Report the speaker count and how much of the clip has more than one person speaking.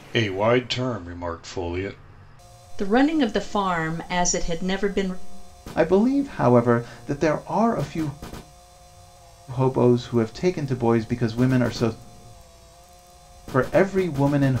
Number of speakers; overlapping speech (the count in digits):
3, no overlap